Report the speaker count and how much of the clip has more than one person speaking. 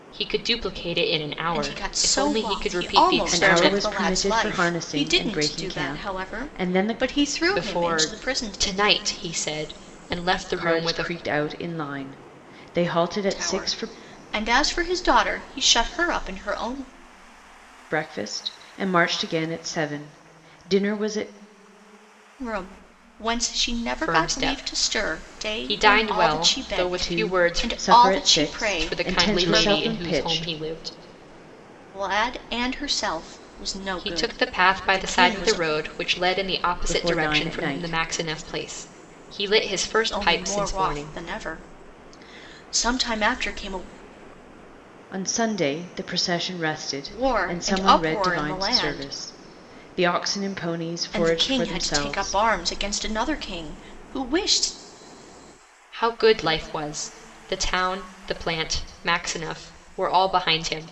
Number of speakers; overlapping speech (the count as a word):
three, about 36%